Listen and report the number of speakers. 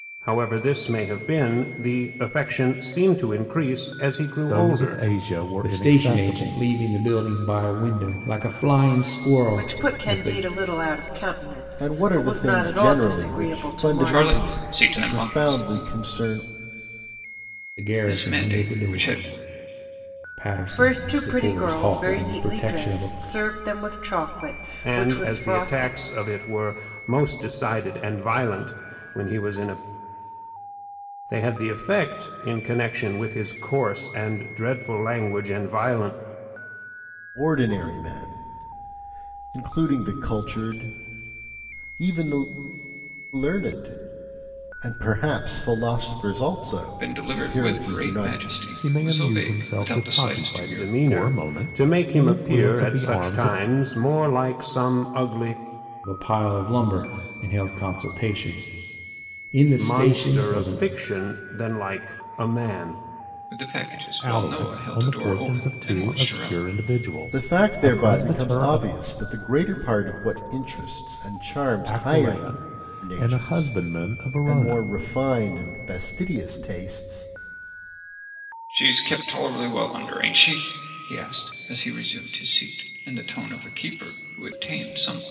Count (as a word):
six